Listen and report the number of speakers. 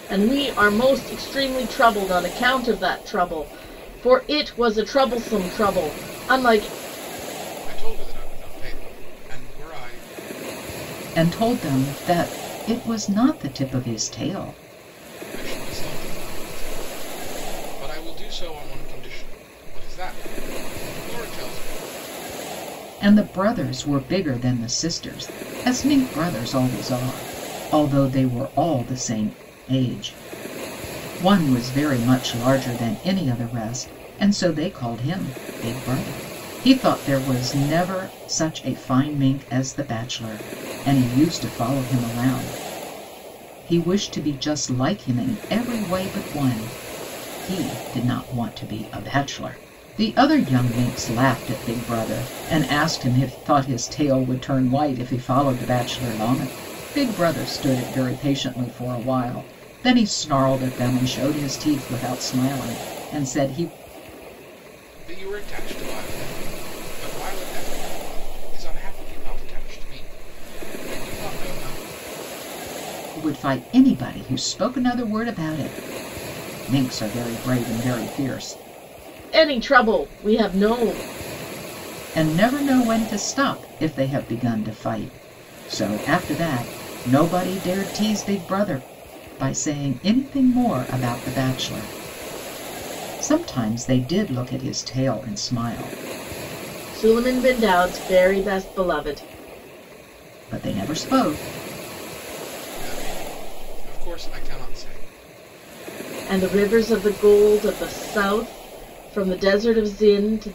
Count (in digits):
3